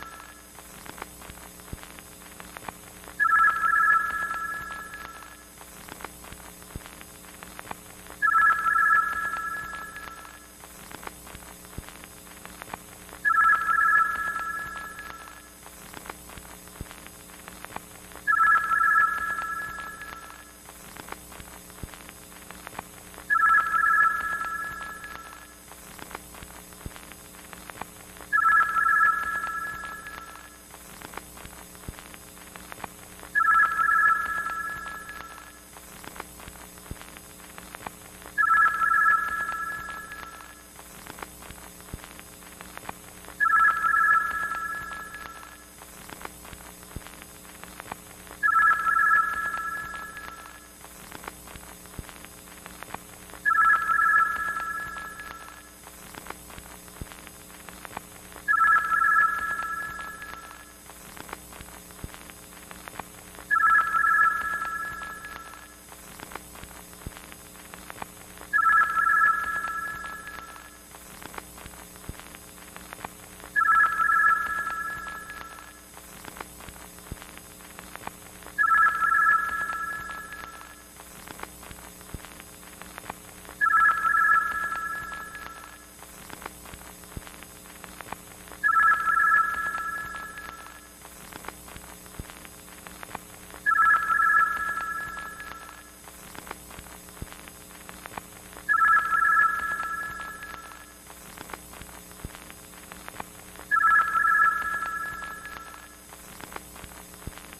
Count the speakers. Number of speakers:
zero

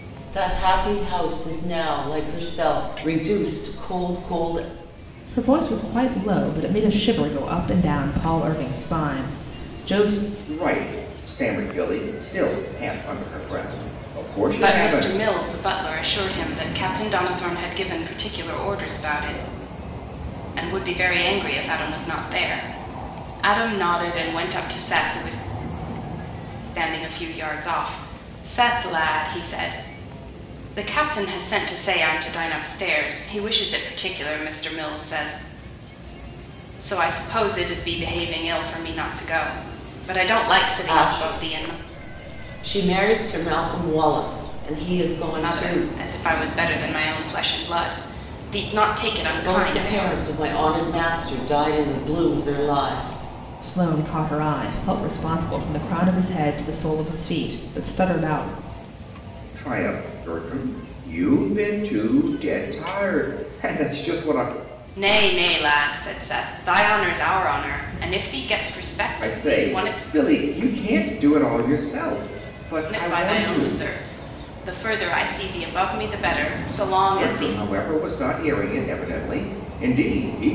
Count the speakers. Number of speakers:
four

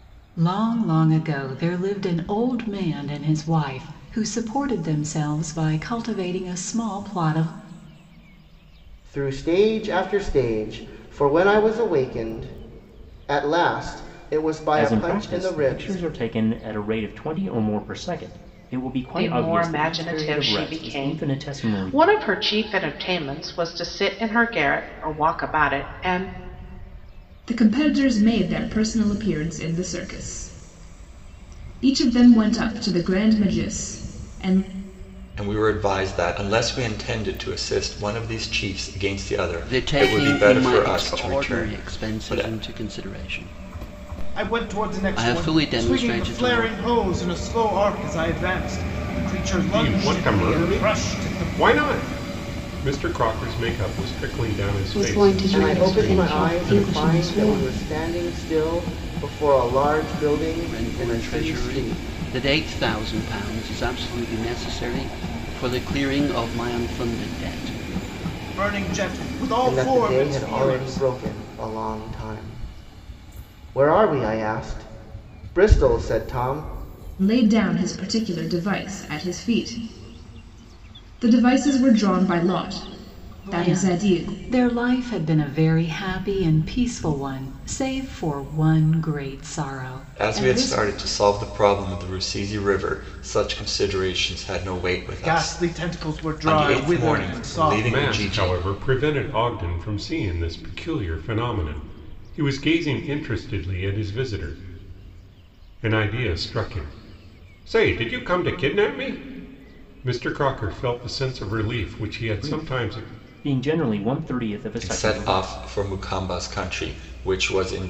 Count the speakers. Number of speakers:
ten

